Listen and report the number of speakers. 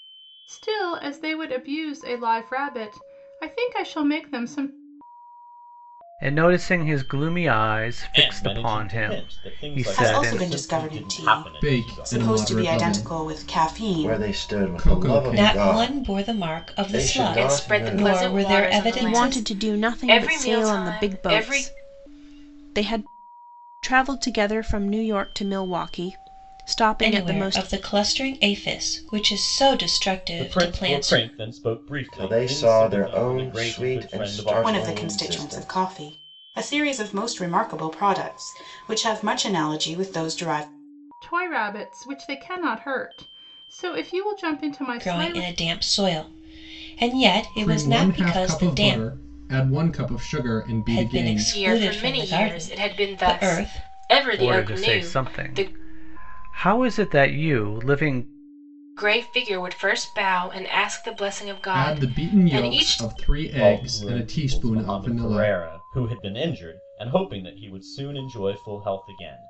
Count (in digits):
9